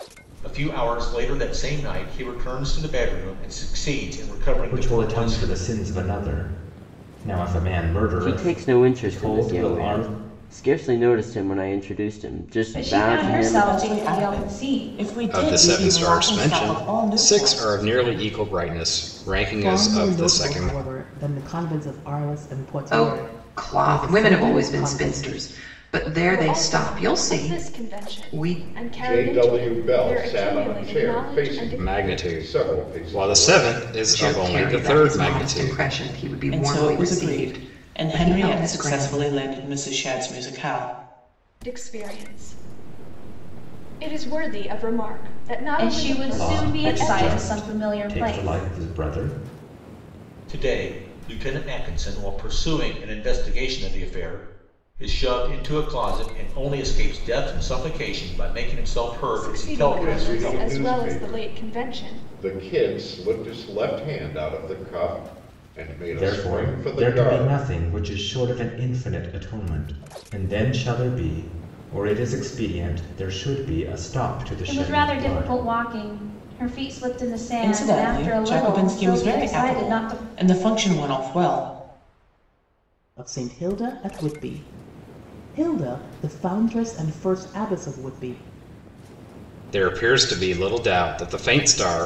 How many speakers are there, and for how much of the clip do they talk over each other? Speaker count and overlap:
10, about 37%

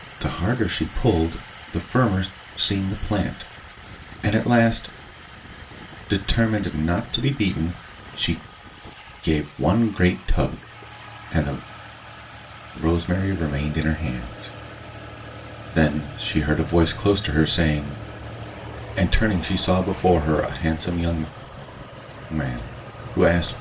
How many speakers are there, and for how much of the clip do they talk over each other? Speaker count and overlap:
1, no overlap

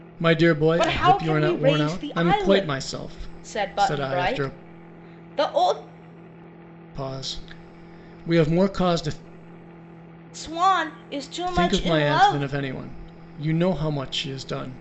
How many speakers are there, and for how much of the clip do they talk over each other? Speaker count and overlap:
2, about 30%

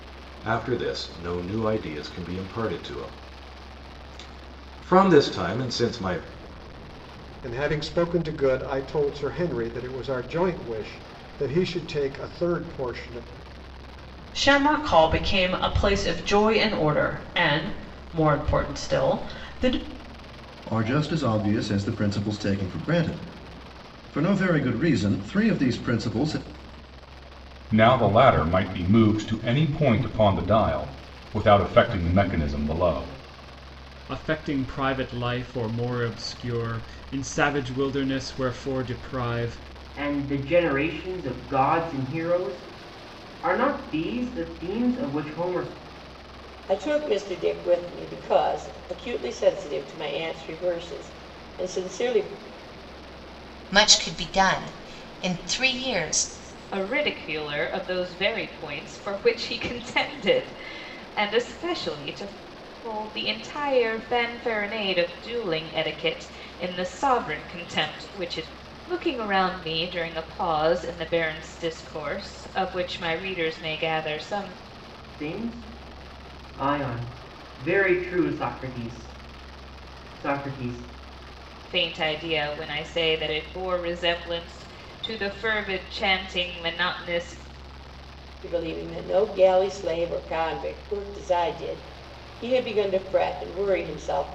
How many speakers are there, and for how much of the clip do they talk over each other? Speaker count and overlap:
10, no overlap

